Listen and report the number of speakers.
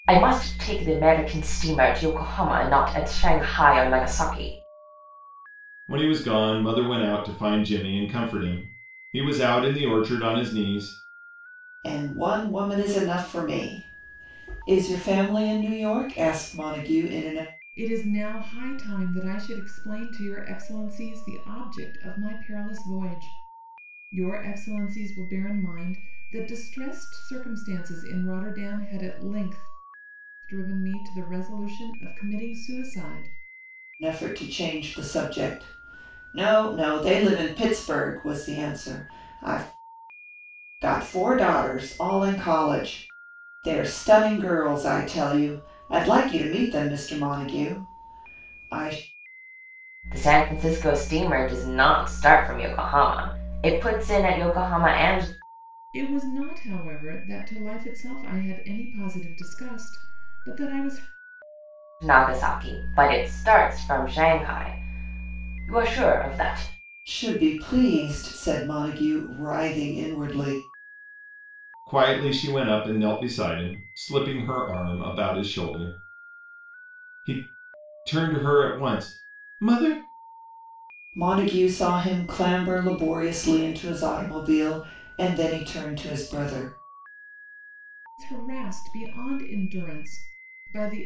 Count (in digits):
4